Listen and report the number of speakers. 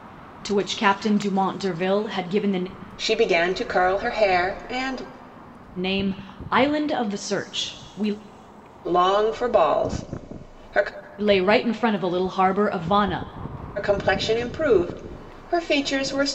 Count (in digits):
2